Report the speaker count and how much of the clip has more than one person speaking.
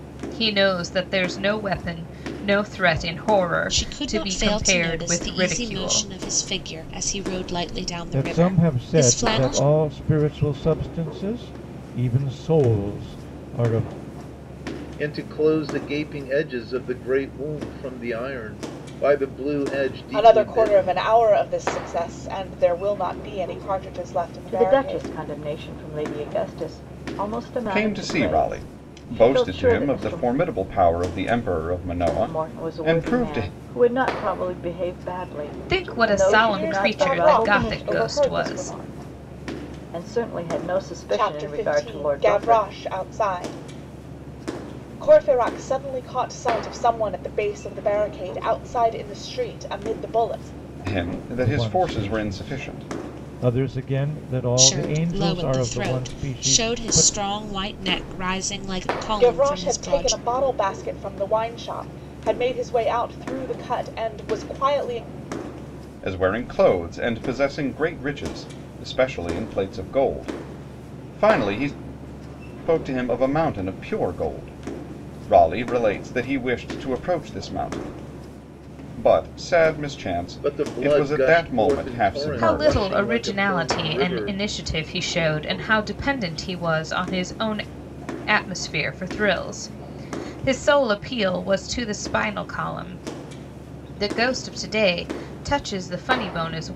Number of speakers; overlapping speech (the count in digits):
7, about 25%